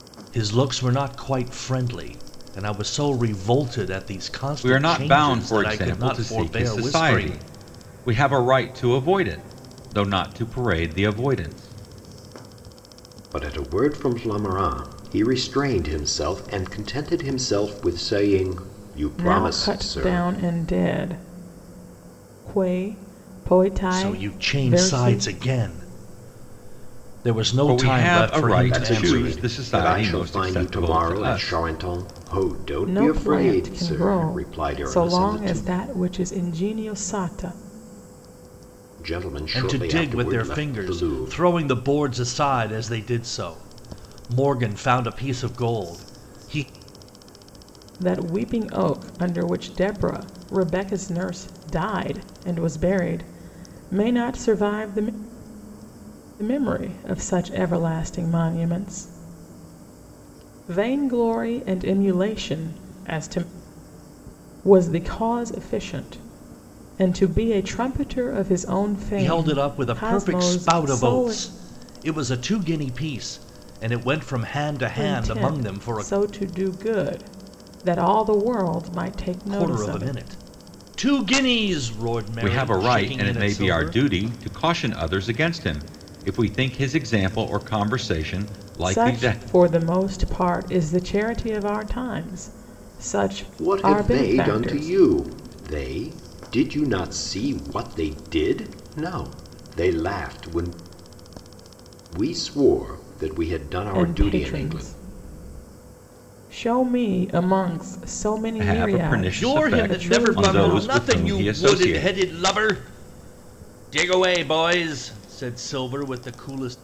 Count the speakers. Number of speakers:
4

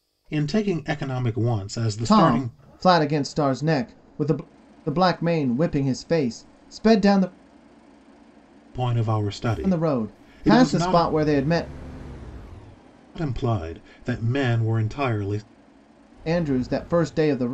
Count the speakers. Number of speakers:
2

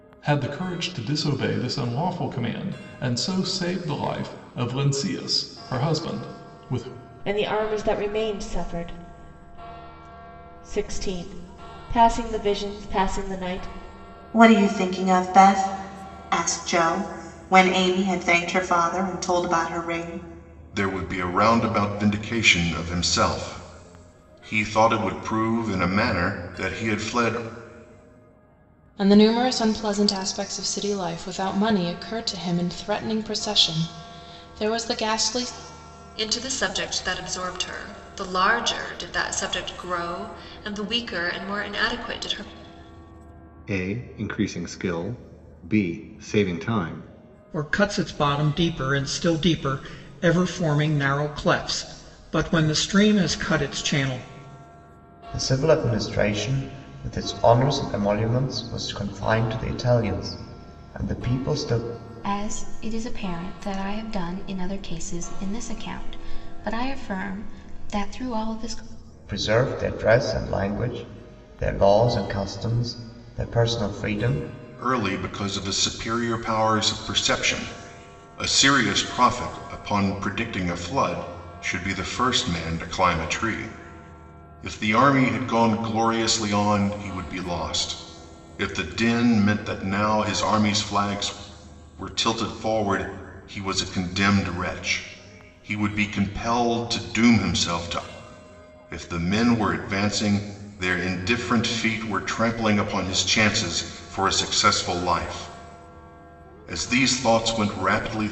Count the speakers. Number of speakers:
10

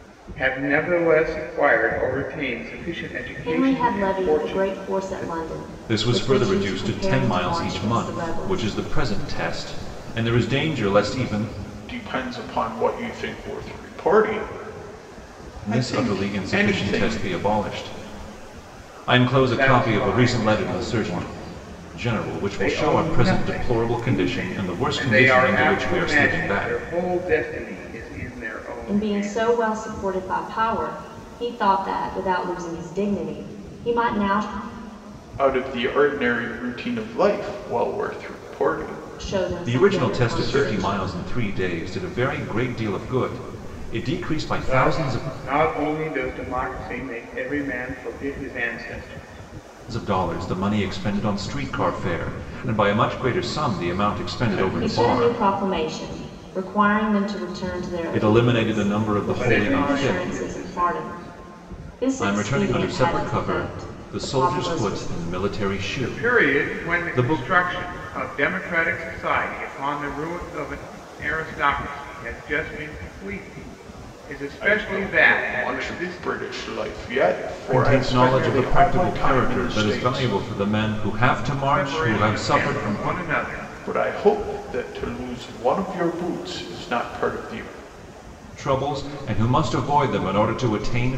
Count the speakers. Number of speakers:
4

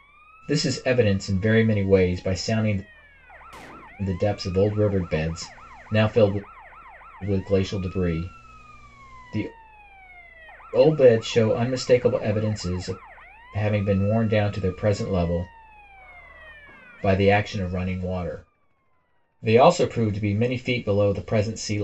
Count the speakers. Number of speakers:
1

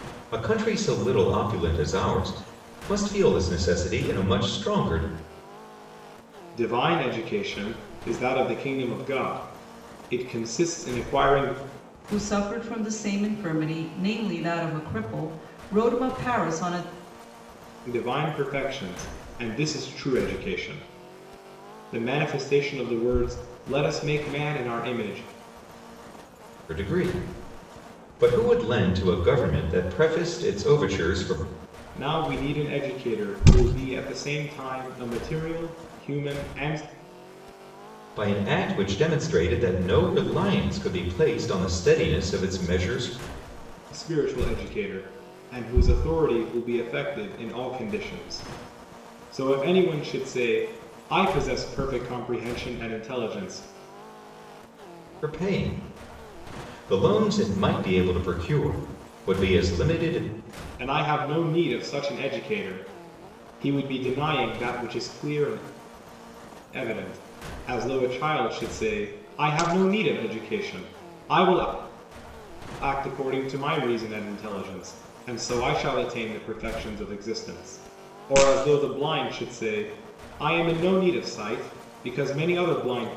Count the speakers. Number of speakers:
3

